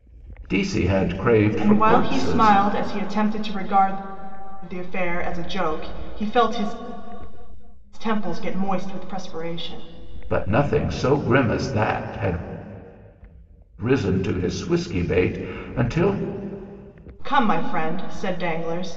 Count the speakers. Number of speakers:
2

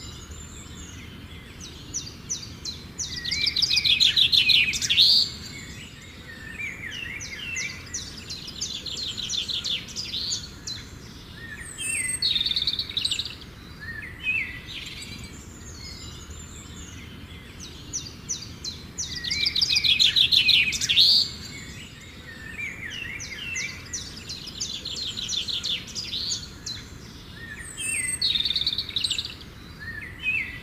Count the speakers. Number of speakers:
0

